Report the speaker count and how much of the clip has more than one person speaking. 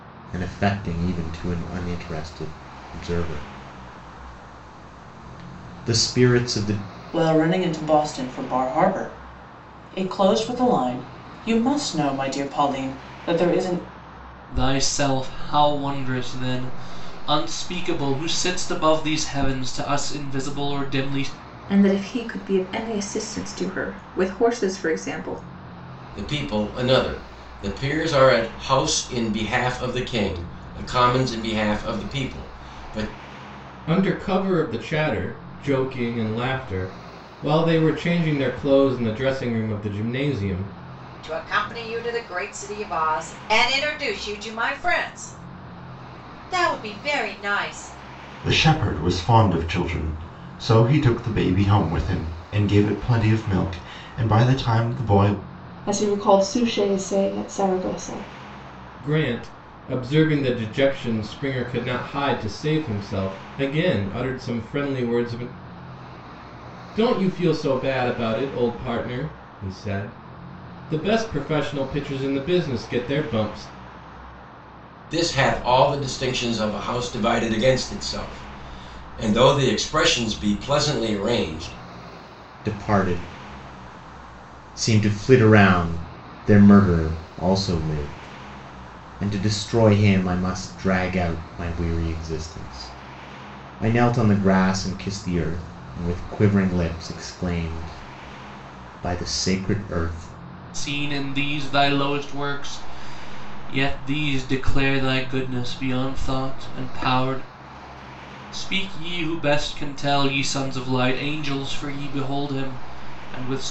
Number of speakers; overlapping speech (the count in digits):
9, no overlap